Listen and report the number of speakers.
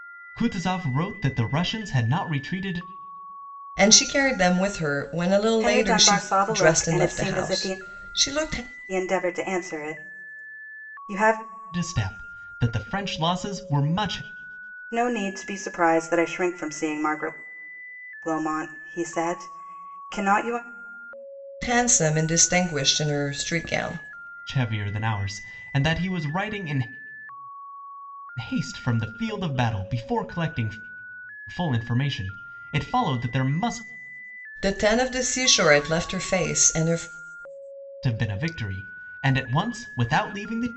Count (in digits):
3